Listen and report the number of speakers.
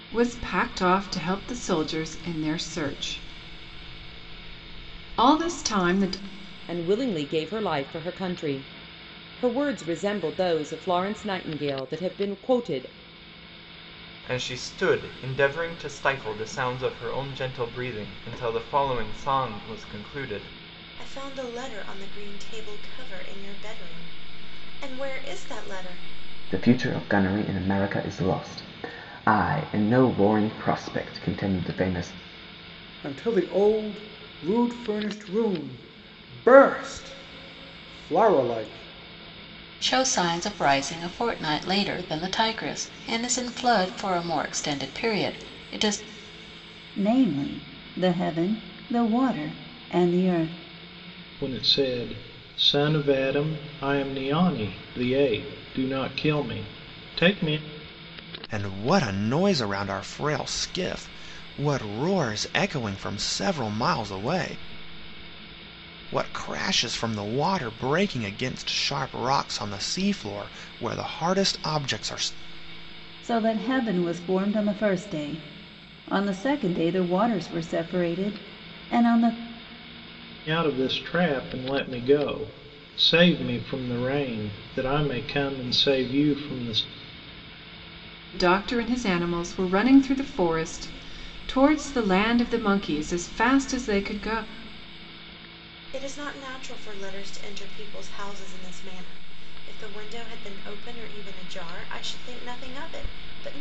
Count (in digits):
10